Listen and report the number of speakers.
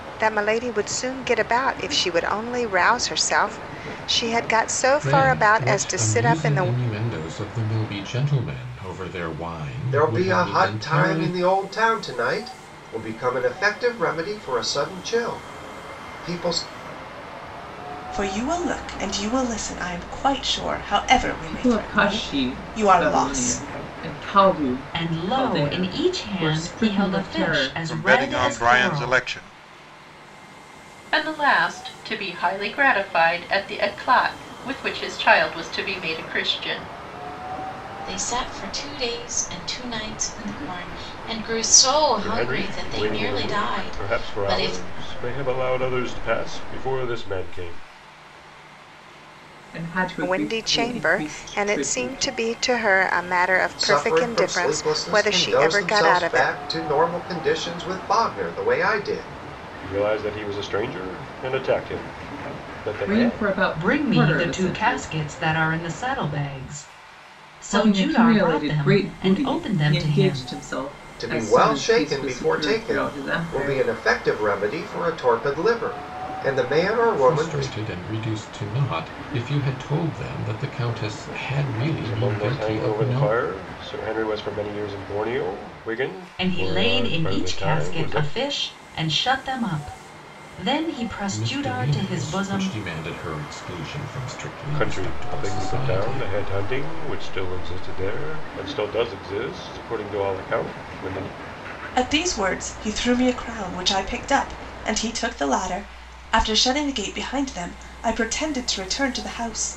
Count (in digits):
10